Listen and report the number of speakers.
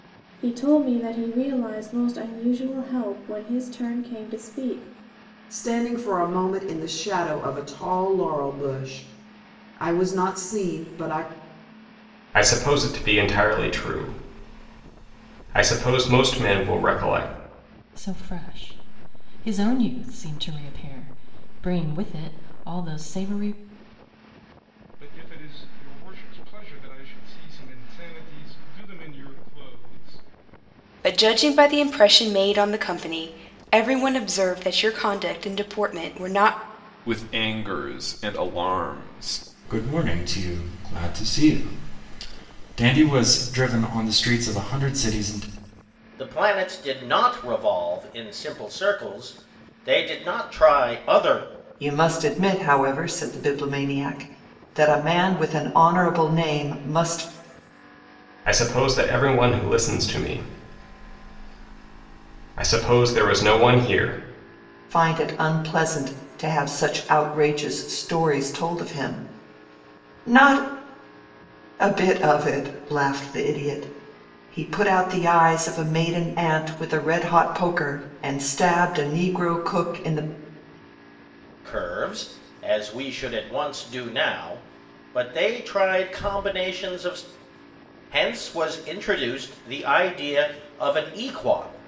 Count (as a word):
ten